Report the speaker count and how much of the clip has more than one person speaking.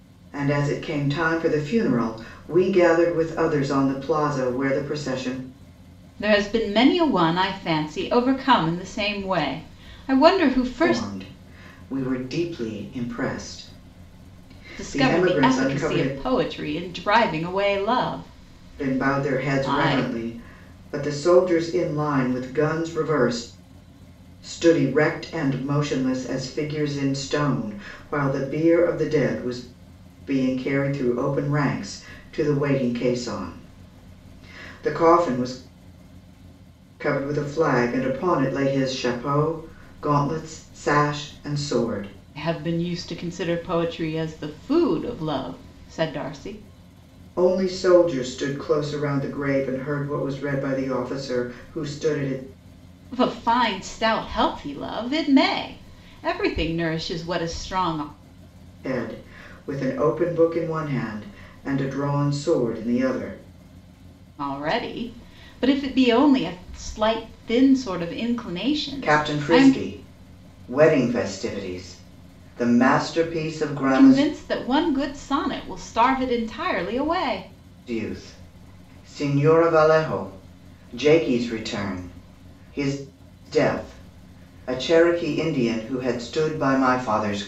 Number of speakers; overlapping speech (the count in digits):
2, about 5%